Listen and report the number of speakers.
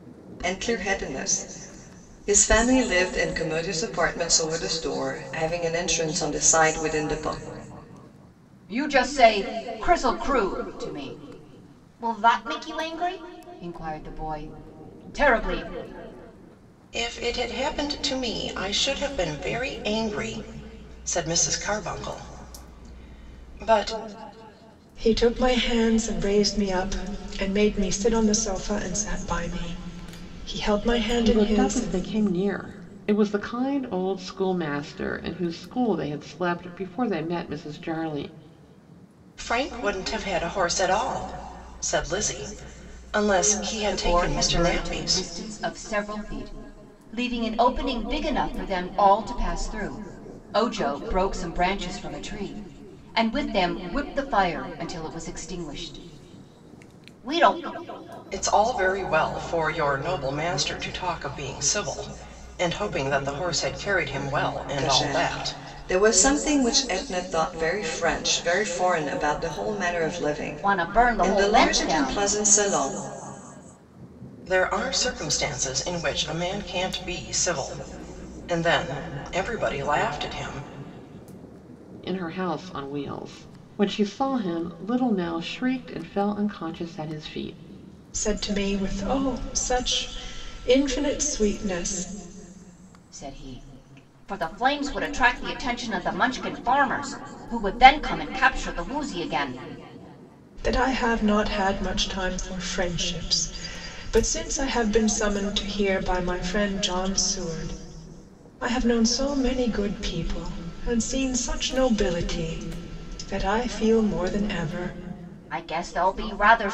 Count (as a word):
five